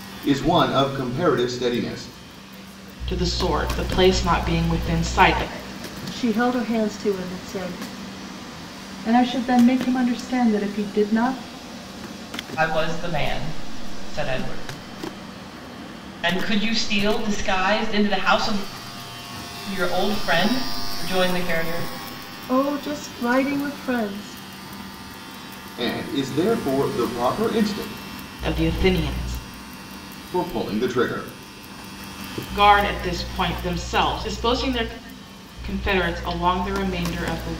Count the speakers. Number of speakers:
five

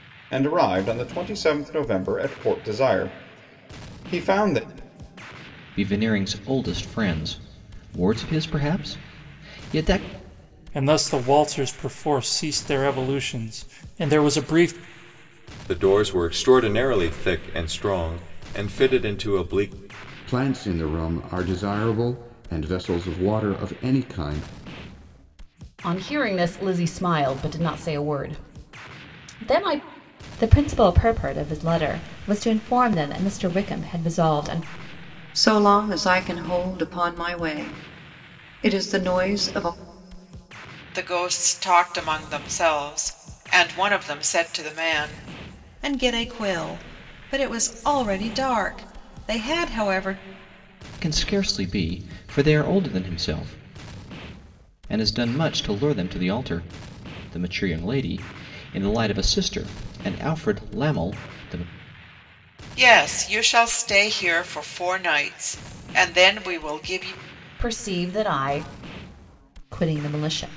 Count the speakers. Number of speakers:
ten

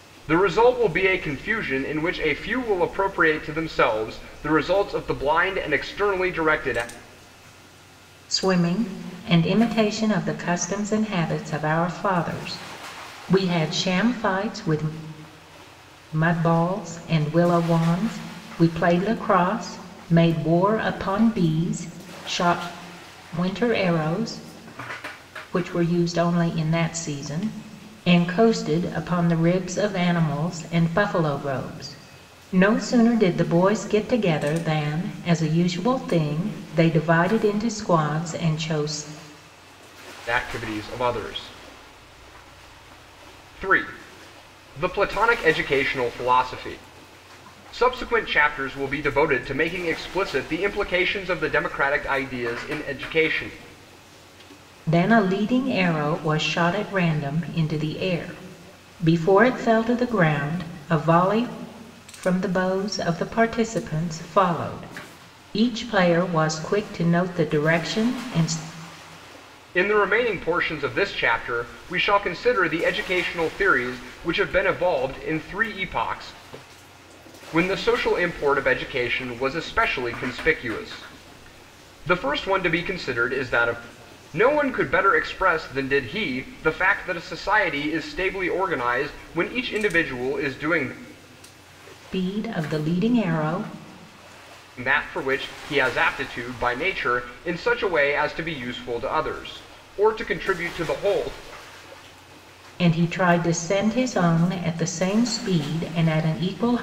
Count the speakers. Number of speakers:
two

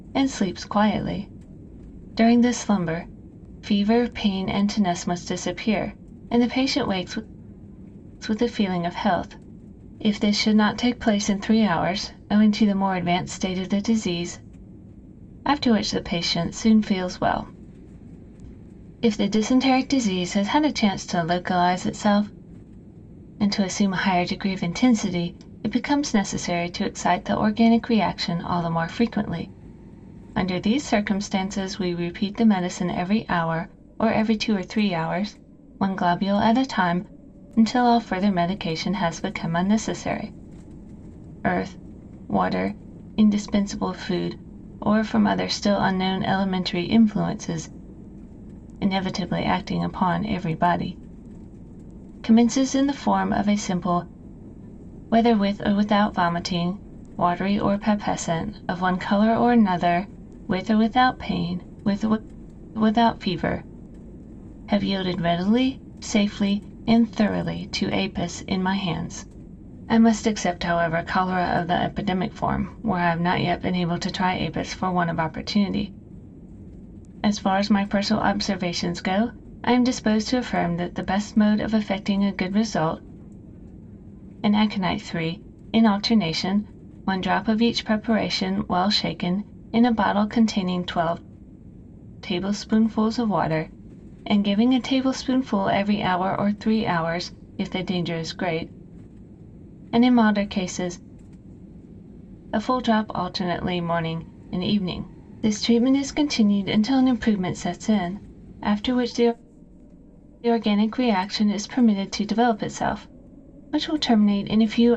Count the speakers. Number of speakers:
one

